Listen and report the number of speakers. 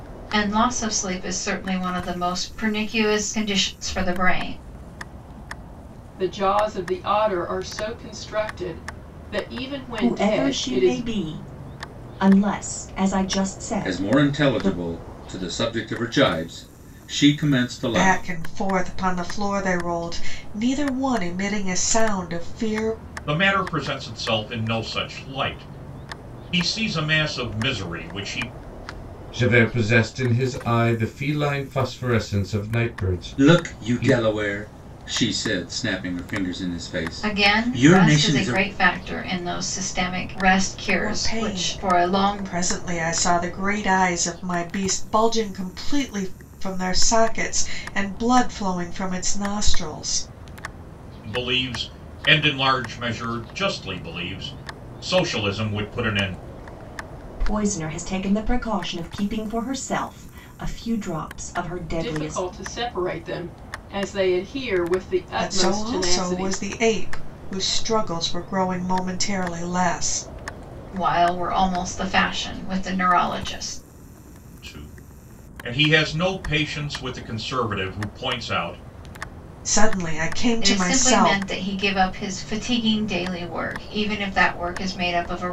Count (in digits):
7